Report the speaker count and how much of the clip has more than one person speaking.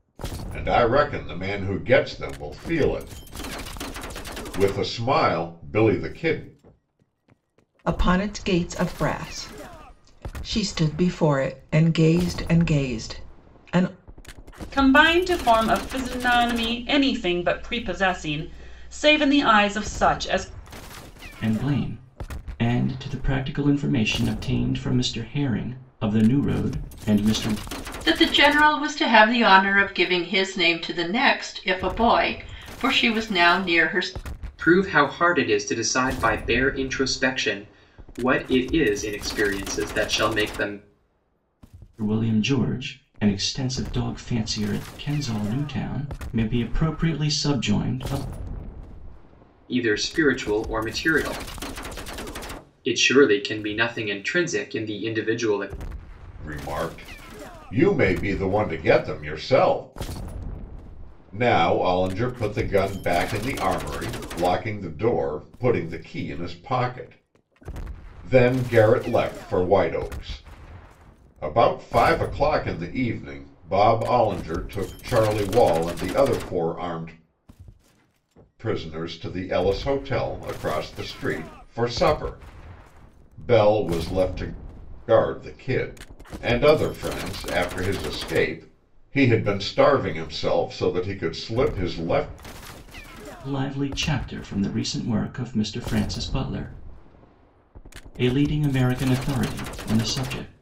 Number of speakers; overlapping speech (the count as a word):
six, no overlap